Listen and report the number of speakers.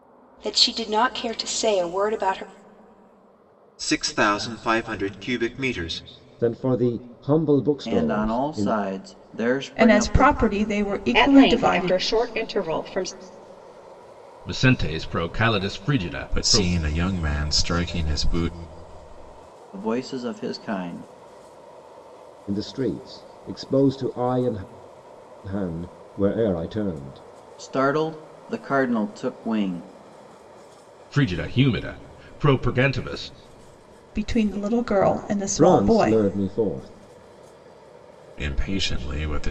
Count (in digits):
8